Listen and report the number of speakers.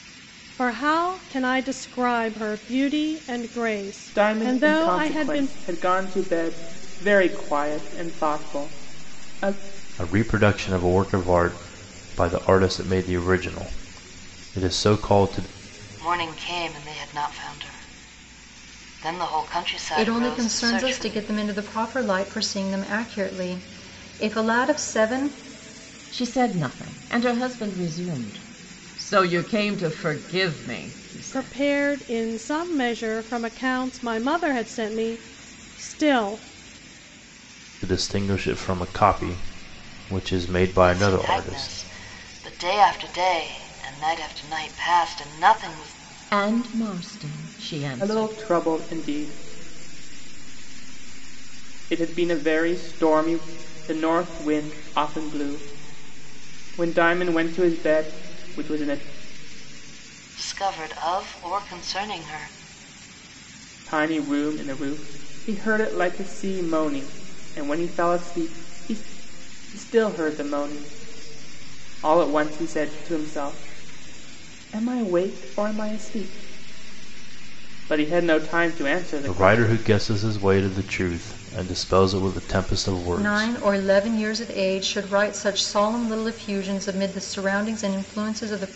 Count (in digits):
6